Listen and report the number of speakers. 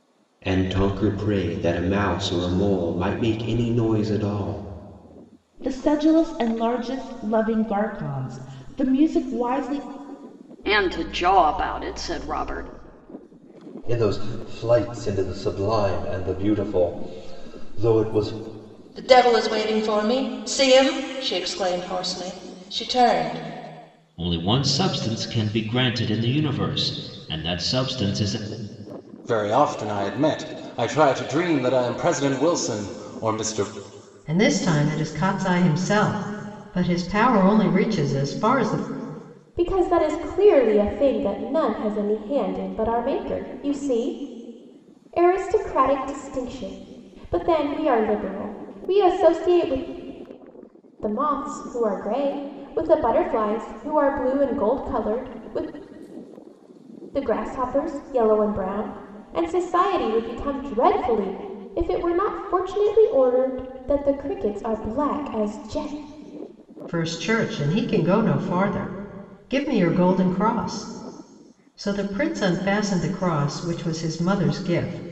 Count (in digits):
9